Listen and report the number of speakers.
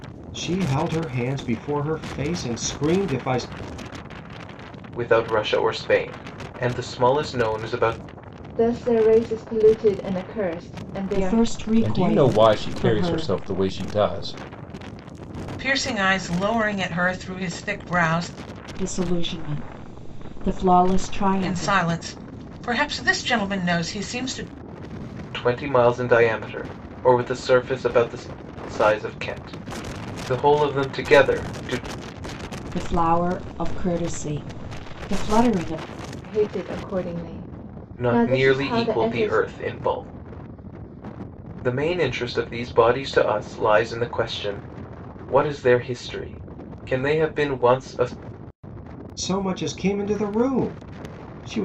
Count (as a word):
six